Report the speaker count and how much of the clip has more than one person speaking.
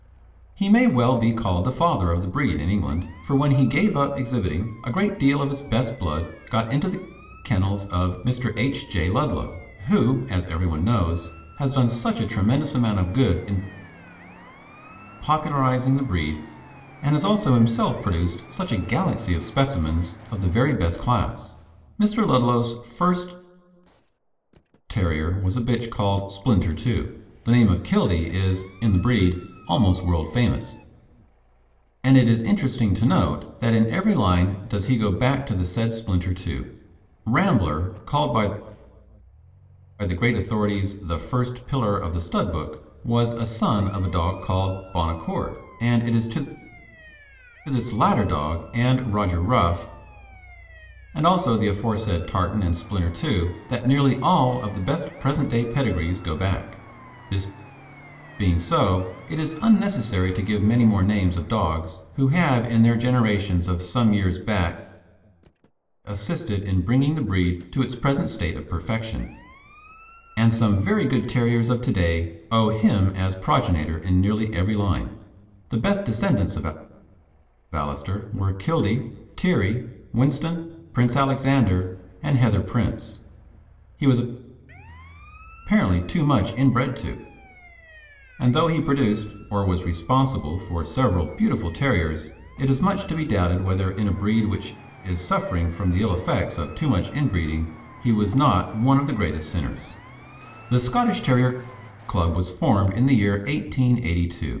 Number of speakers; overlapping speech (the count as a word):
one, no overlap